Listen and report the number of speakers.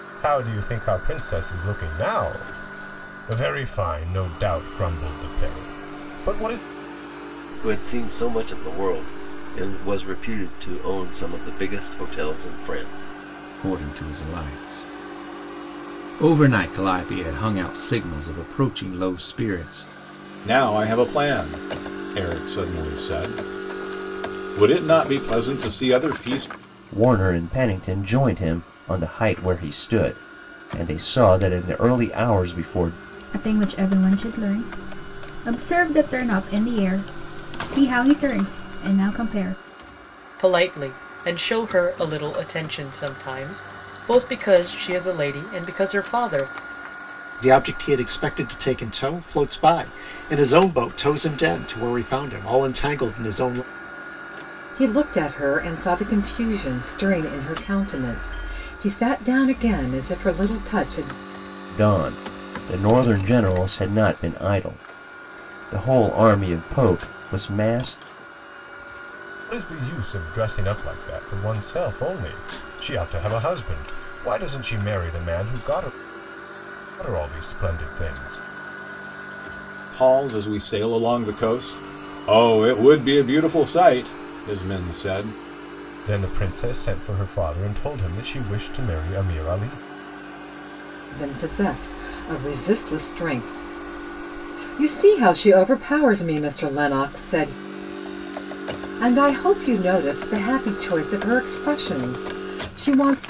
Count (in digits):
9